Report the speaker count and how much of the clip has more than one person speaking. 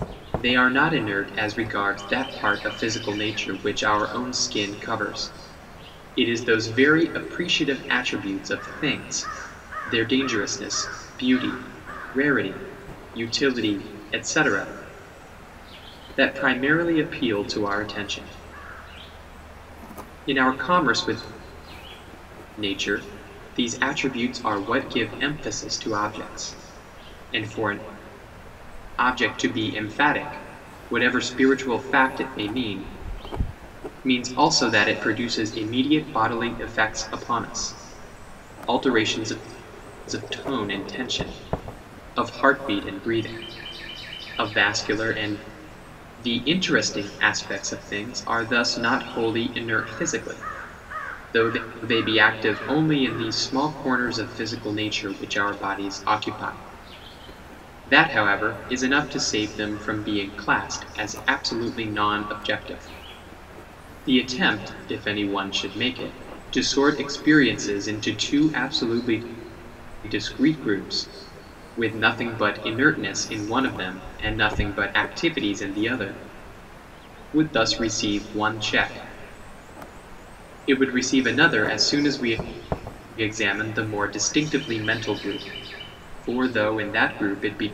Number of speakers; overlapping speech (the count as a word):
one, no overlap